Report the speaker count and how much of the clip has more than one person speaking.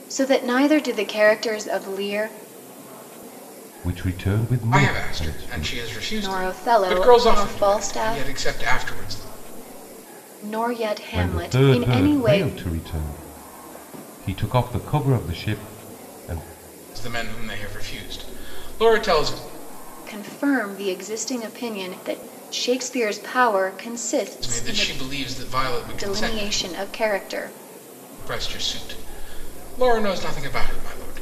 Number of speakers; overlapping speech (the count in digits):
3, about 18%